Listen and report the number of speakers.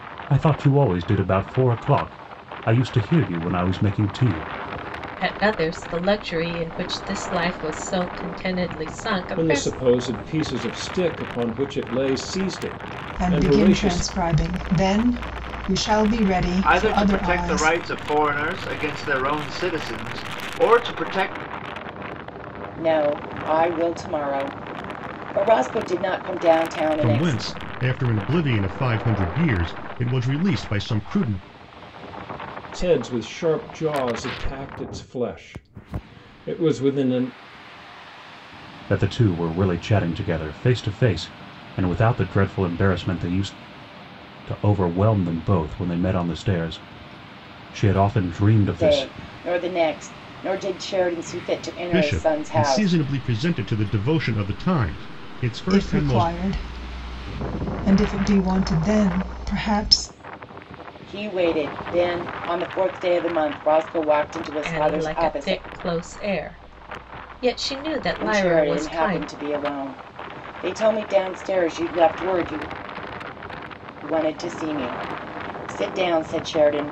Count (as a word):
seven